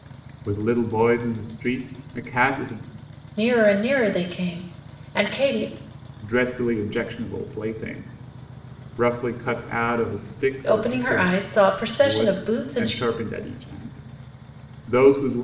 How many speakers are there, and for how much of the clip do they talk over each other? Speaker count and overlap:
two, about 10%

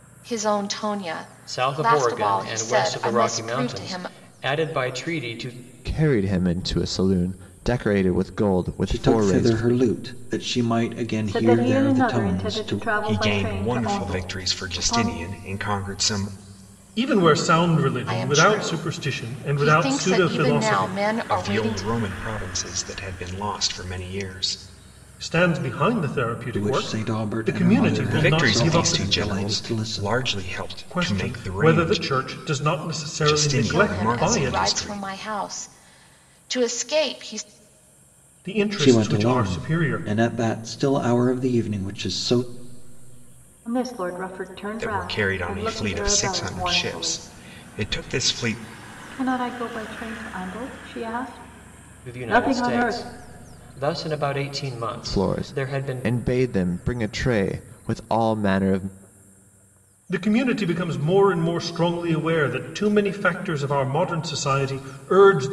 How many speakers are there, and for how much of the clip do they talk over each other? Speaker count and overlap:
seven, about 36%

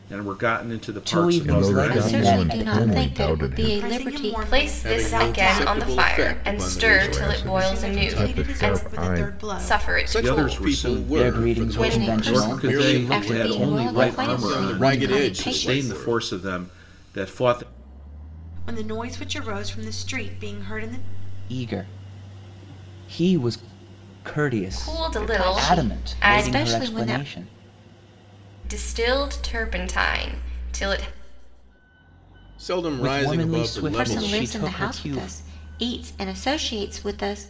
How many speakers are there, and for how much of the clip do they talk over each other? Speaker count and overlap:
seven, about 54%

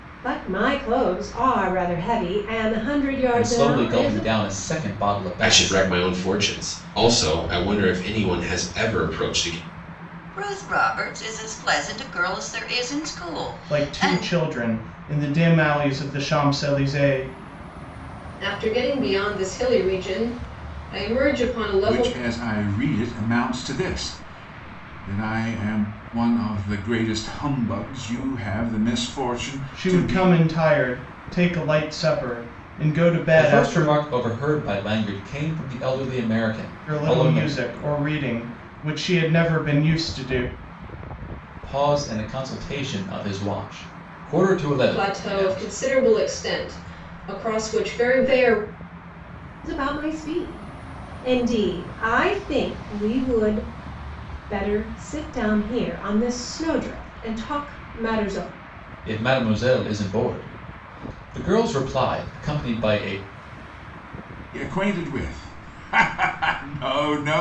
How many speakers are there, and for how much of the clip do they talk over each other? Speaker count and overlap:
seven, about 8%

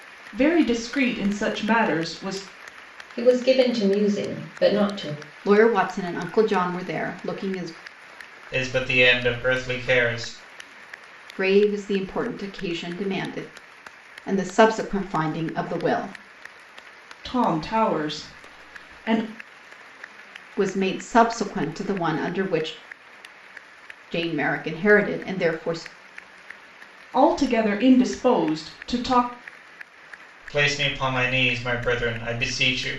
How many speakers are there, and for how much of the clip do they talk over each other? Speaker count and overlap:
four, no overlap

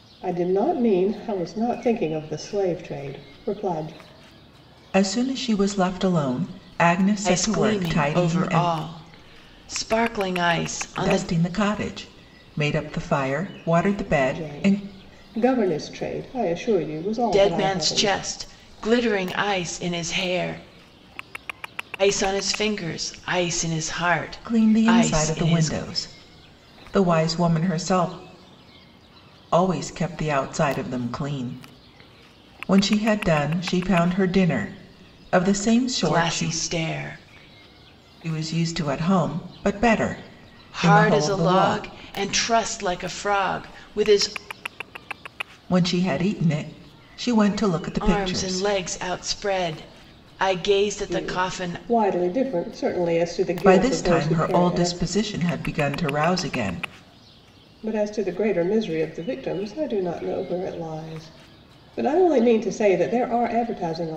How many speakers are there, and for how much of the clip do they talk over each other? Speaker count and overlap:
three, about 14%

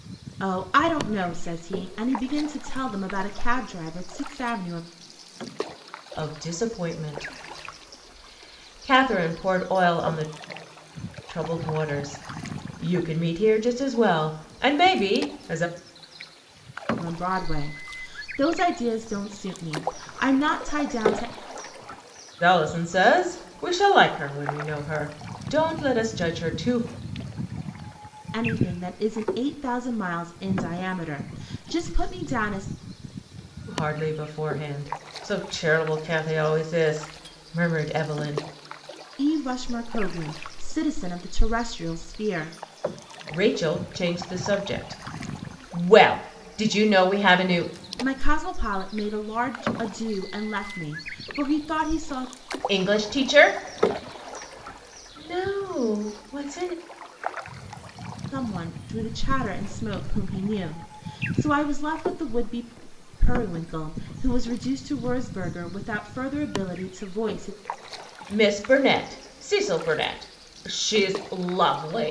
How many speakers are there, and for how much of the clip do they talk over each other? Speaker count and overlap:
two, no overlap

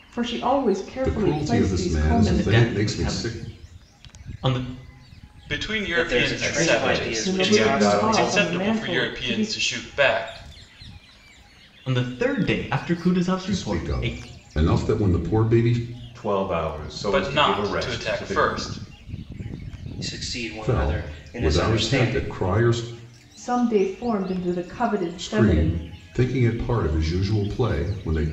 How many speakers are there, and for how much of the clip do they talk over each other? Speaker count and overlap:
six, about 38%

